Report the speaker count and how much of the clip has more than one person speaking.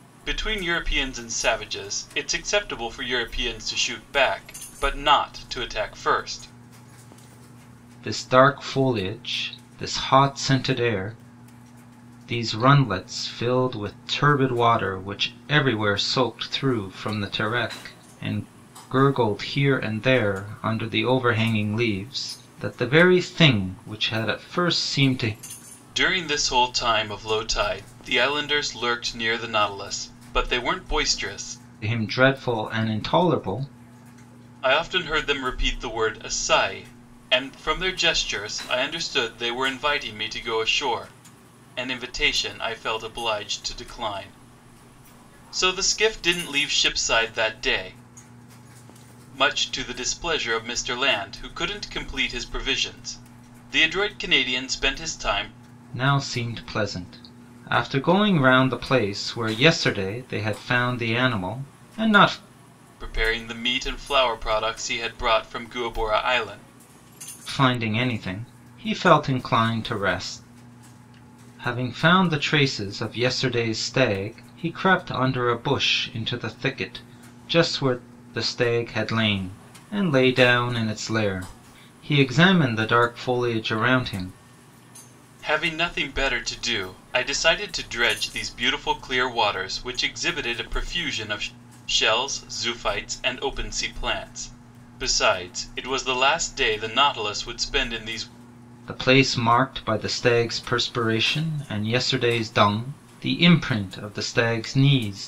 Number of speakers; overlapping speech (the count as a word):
two, no overlap